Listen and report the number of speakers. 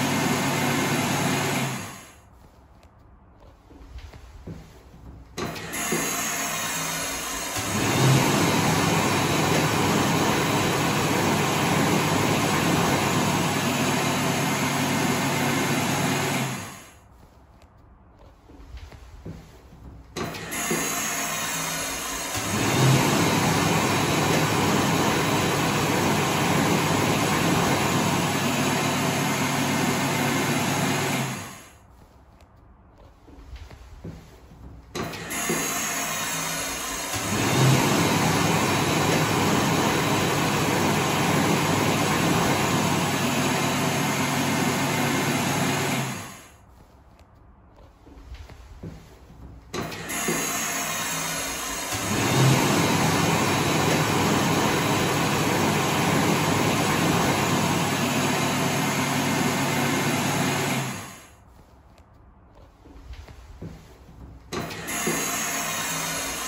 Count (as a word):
zero